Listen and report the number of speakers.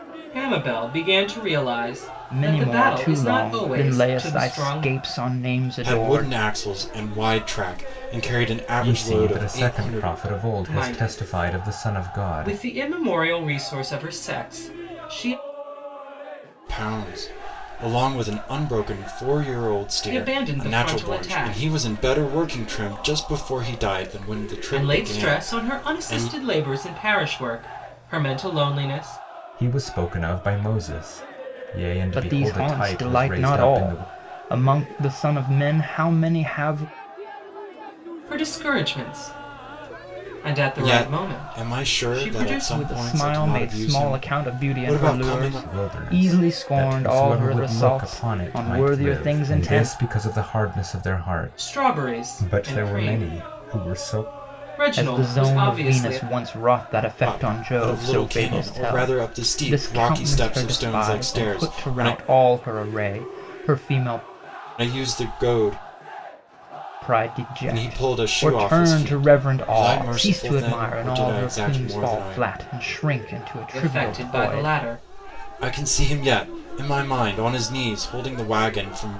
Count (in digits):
4